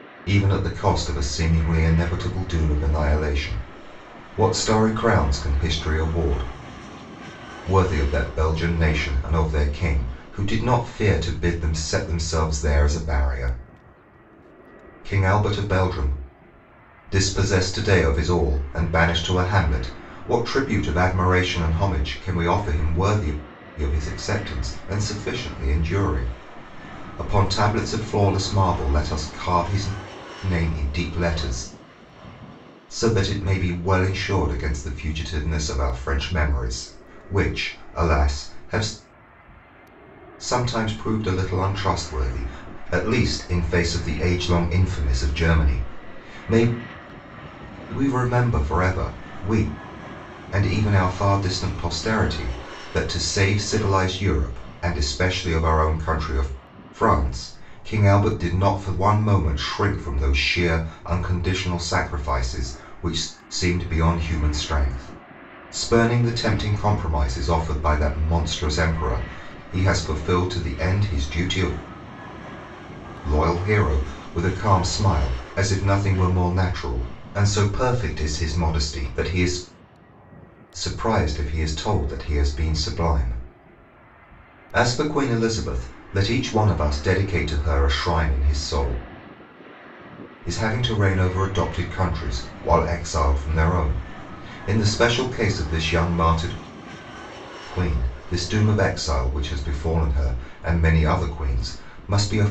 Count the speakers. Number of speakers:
1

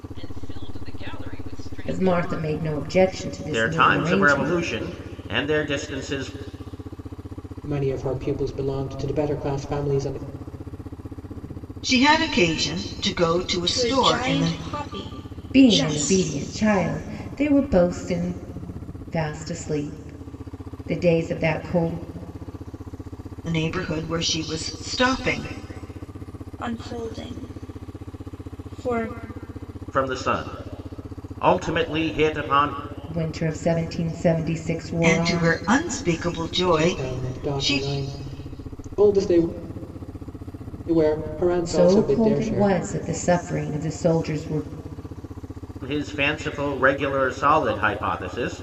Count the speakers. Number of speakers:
6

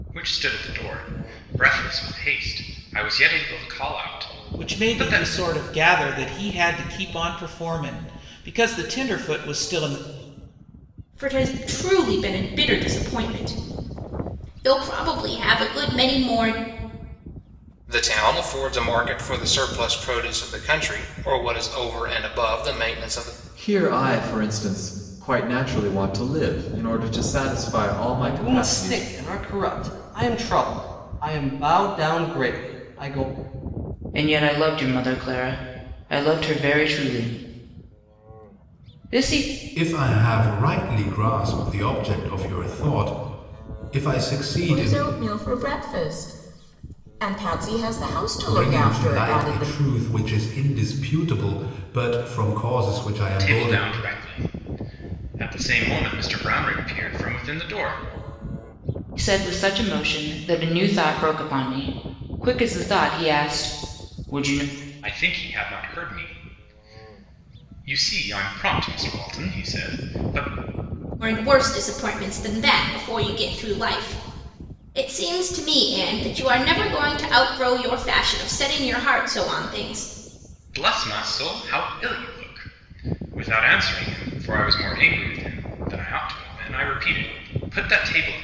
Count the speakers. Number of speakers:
9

